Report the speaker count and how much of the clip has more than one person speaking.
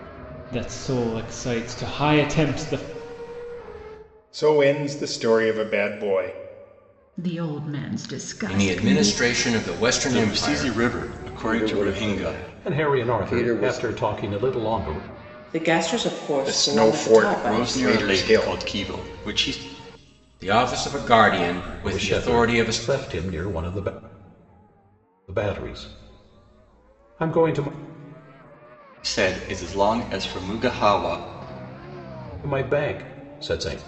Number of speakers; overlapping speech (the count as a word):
eight, about 20%